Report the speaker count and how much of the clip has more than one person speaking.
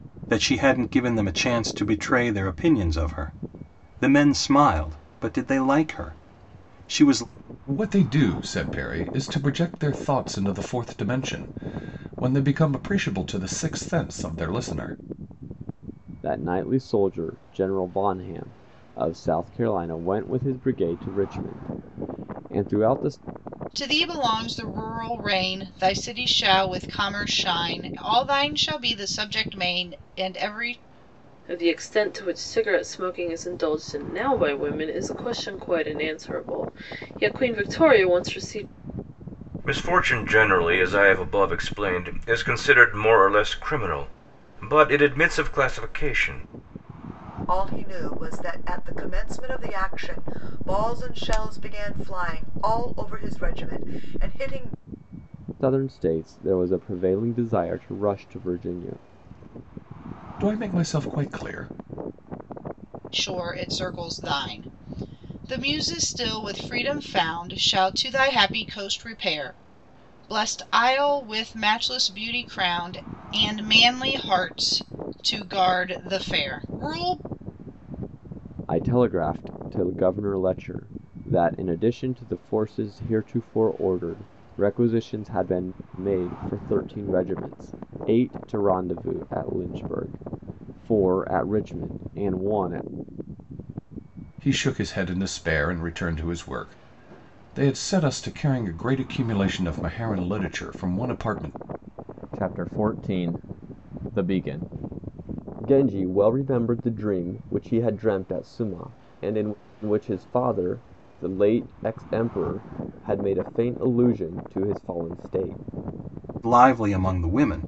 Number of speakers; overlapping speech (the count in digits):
7, no overlap